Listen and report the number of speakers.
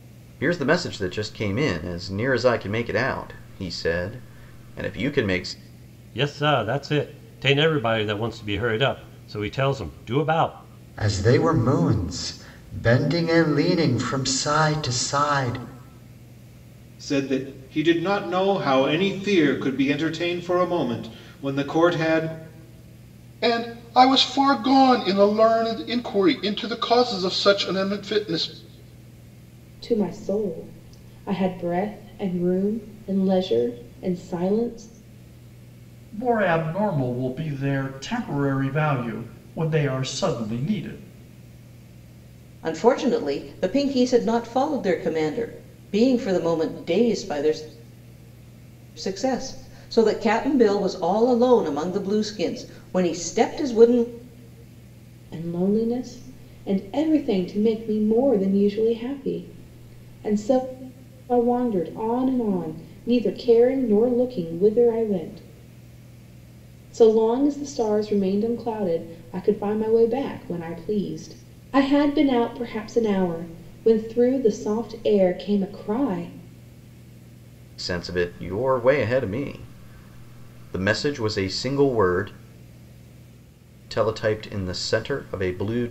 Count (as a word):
eight